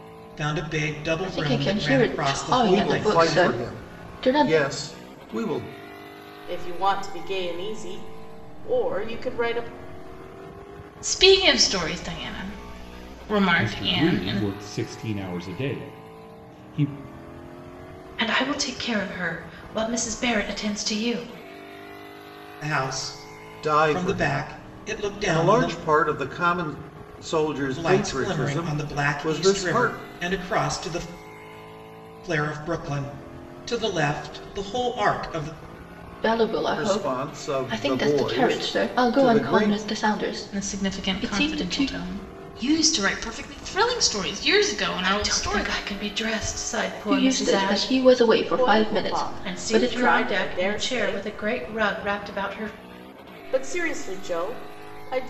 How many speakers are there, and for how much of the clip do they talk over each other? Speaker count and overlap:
7, about 32%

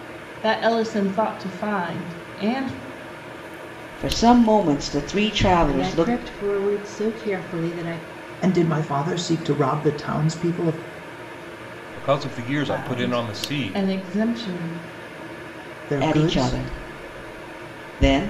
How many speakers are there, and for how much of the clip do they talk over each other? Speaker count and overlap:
5, about 13%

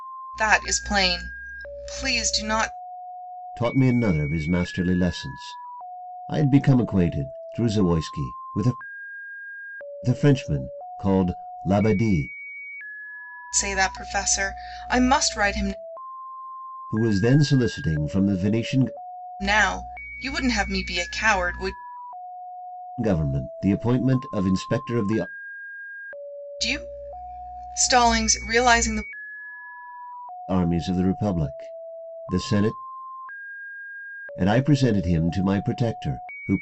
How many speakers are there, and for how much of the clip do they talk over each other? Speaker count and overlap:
2, no overlap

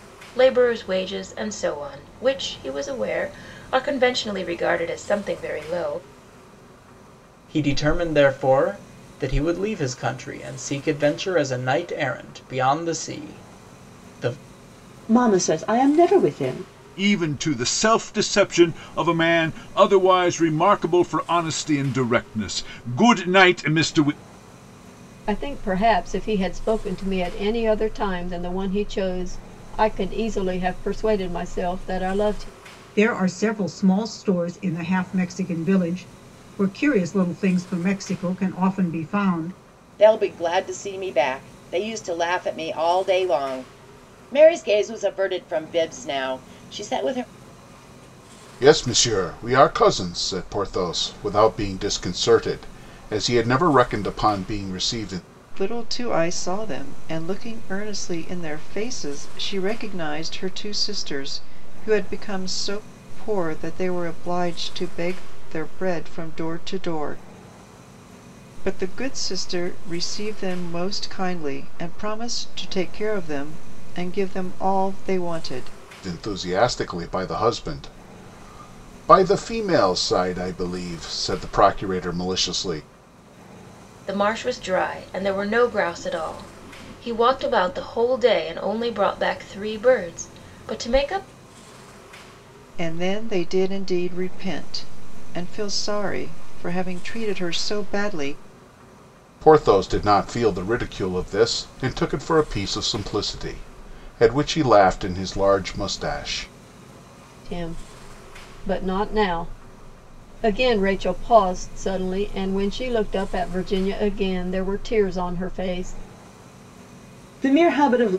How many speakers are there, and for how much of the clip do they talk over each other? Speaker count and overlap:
9, no overlap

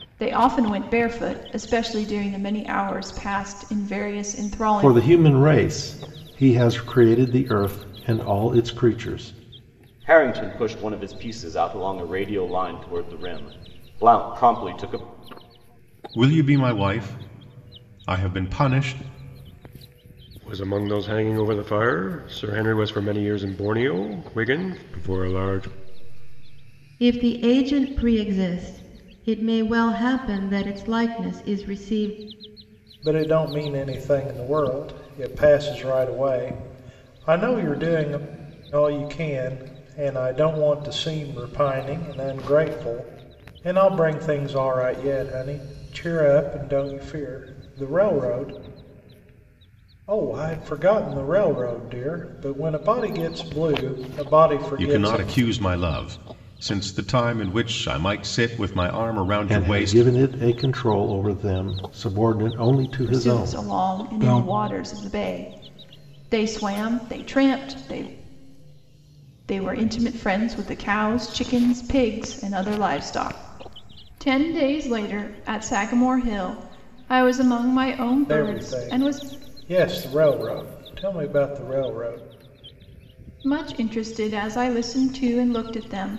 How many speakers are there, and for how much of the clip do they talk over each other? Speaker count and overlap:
7, about 4%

